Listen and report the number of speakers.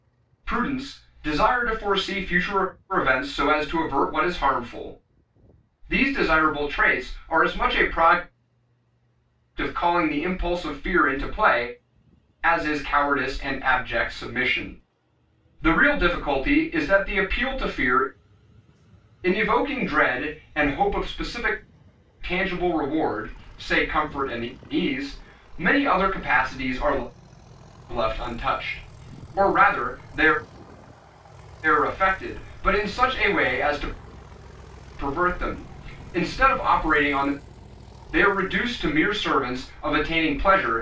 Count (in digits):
1